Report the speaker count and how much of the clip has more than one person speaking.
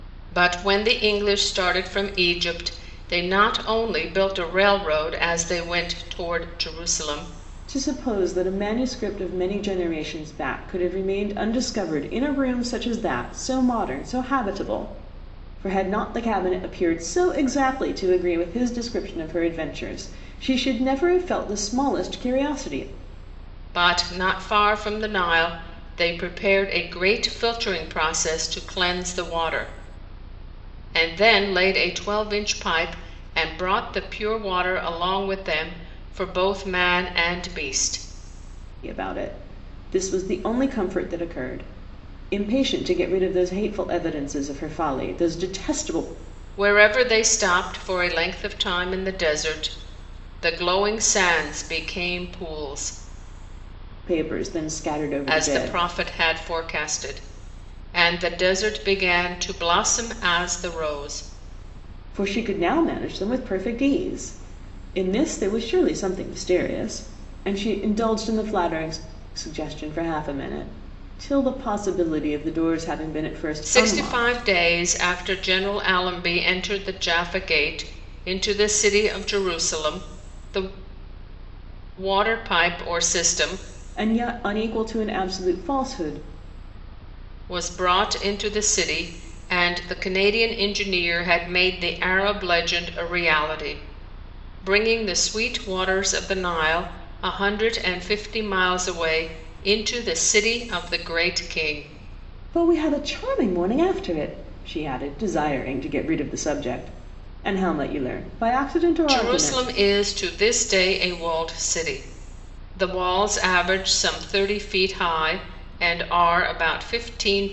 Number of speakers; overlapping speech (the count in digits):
2, about 2%